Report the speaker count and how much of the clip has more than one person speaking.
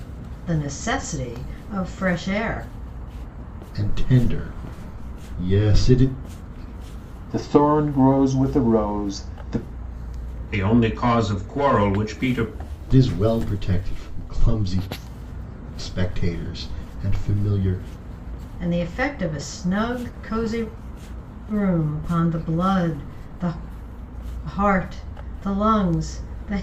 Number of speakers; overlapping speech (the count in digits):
4, no overlap